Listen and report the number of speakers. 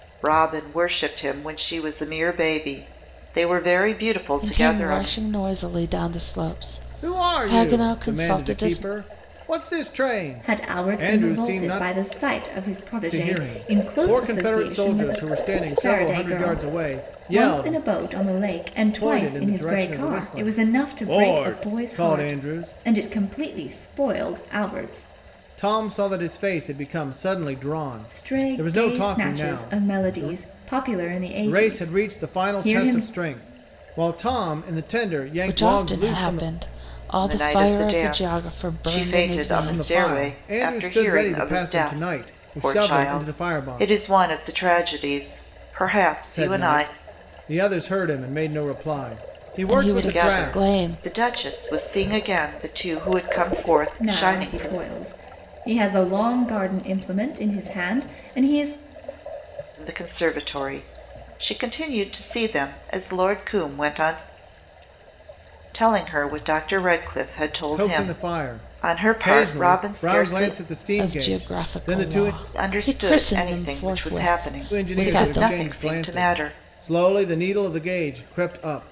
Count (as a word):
four